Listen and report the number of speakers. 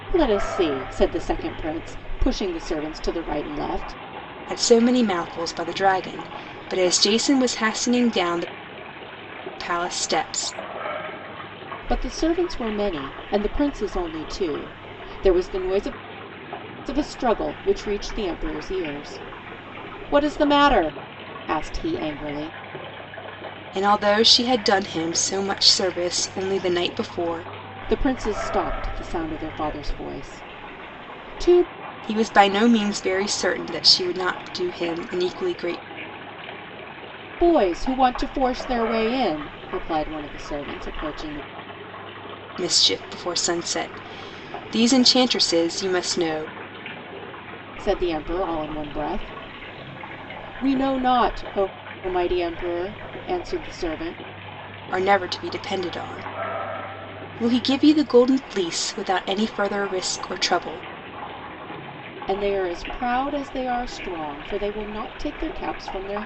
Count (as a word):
two